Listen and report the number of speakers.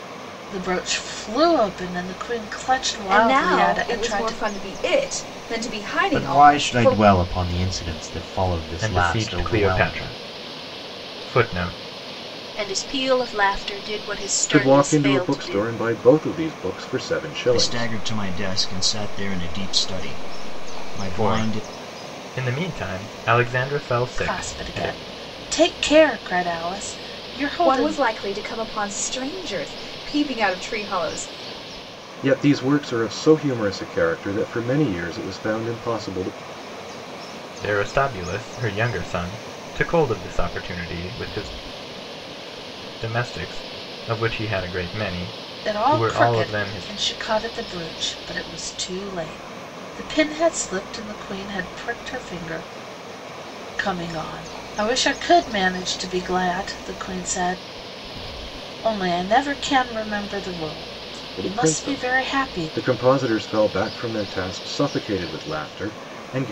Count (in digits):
7